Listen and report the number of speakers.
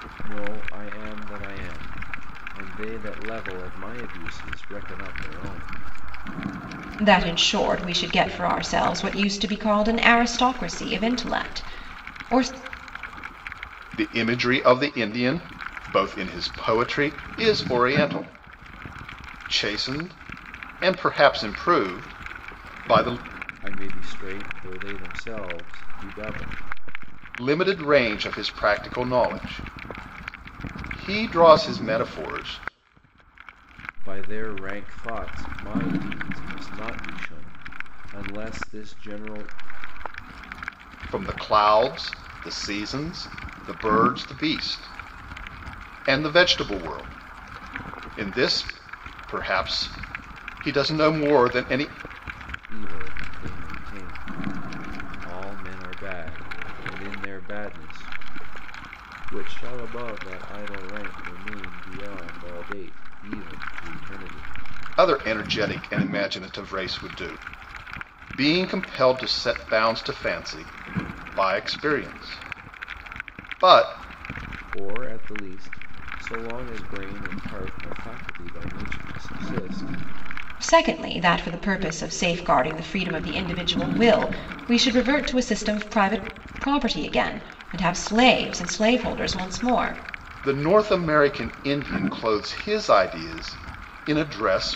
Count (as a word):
three